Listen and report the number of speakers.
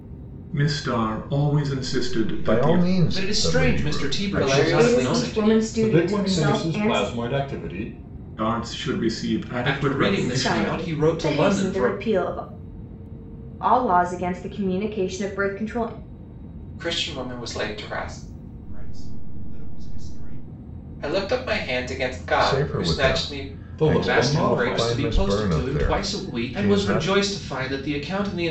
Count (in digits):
7